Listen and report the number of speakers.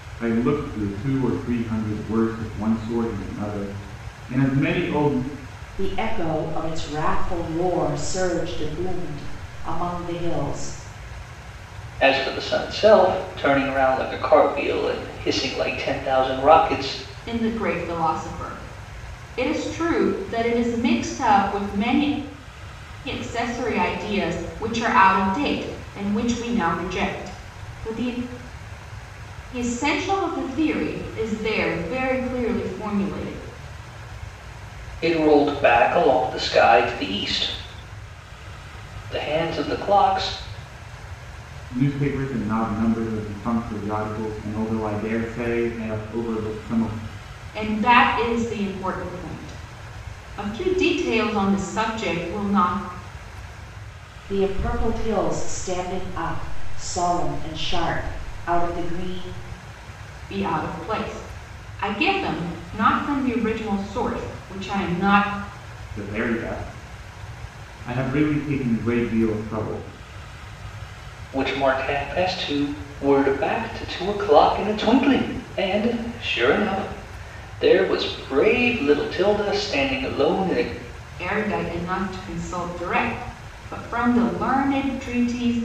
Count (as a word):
four